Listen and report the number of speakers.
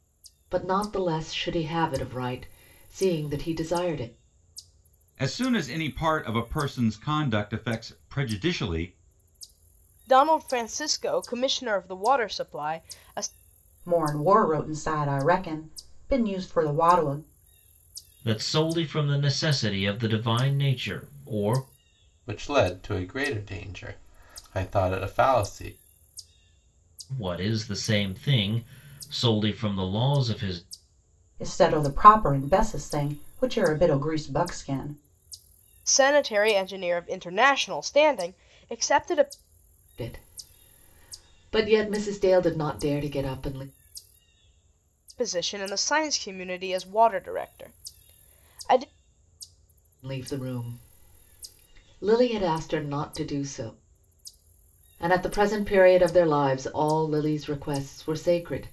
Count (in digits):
6